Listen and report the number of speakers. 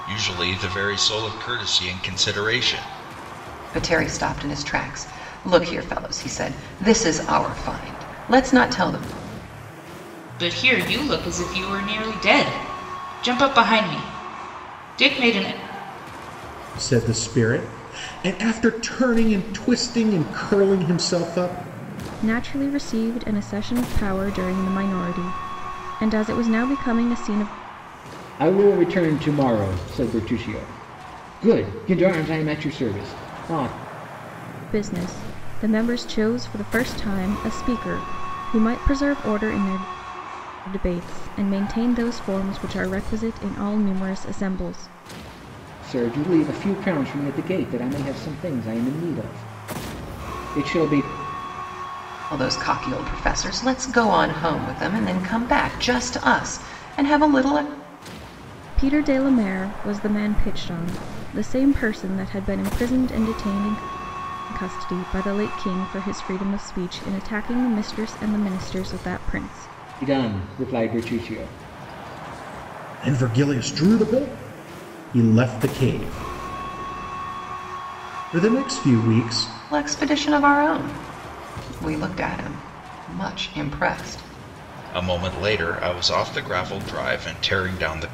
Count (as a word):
six